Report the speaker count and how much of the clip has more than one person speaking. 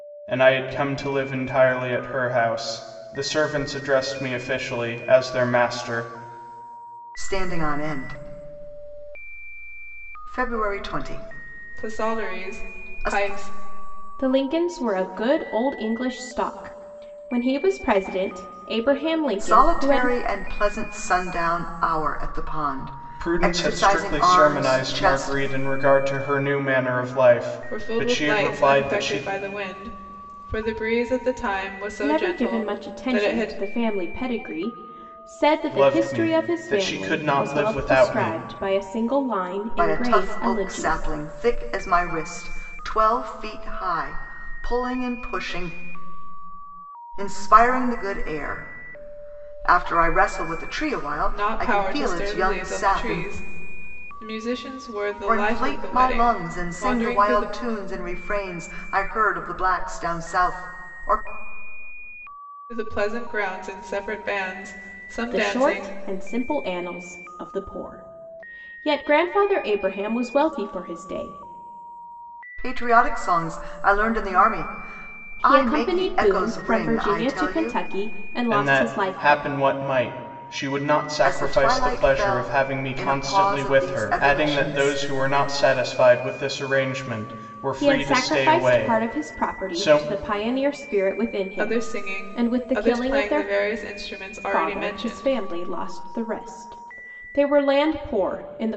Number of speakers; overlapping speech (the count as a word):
four, about 29%